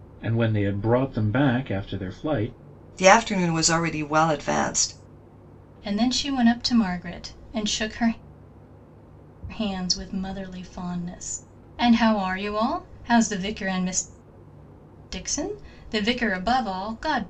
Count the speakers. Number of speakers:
3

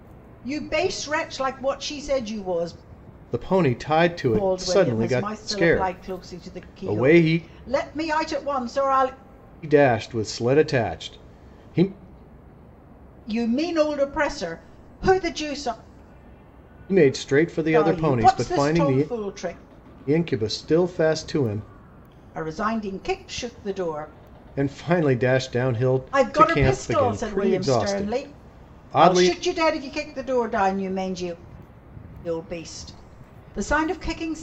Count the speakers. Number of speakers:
2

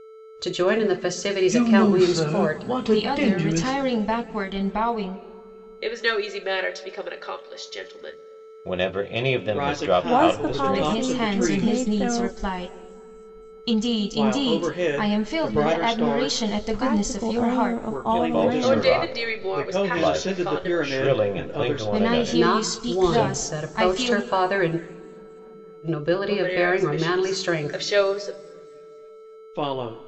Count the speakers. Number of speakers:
7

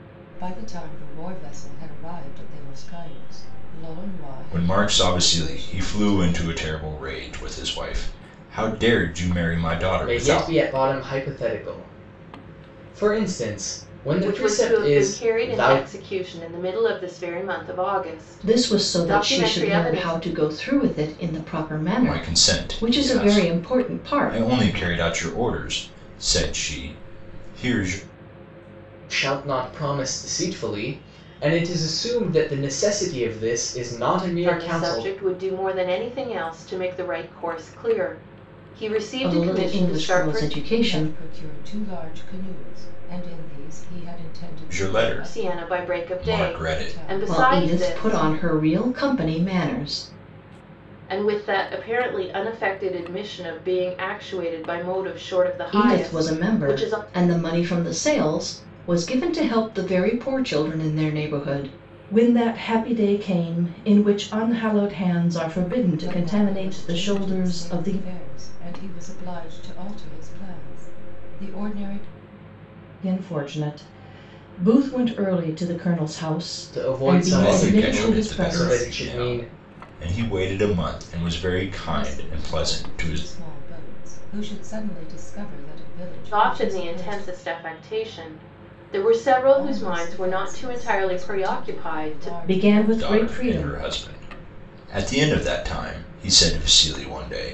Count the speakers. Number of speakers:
5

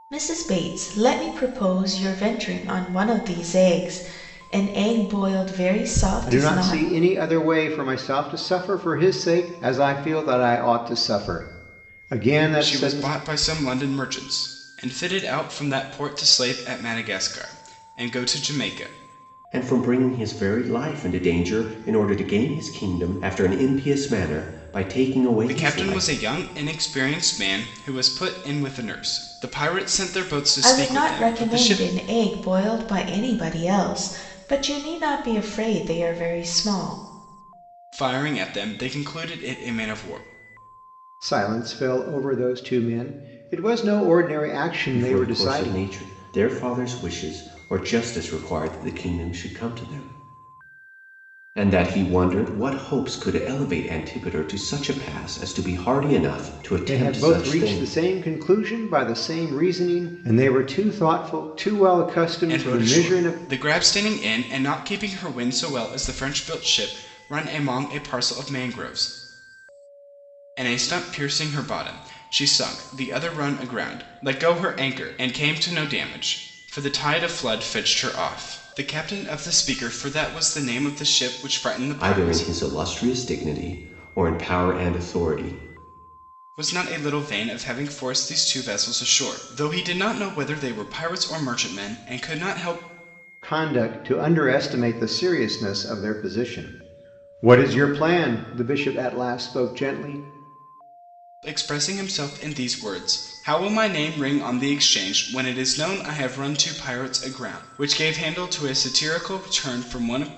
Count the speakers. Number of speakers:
4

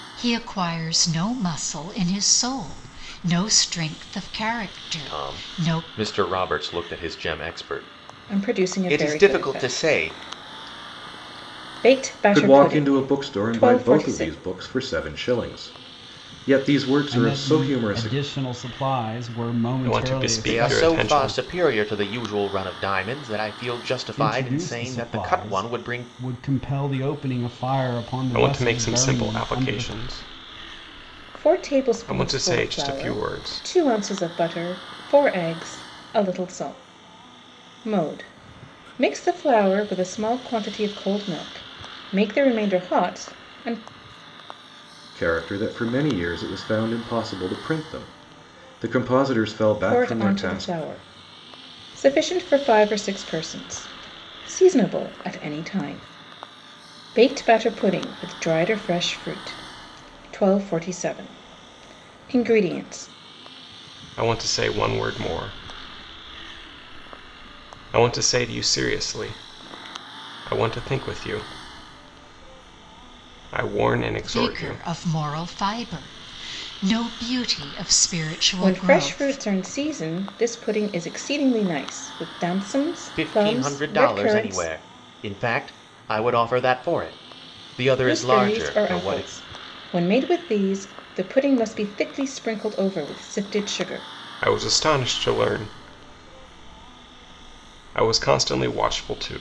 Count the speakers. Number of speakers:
6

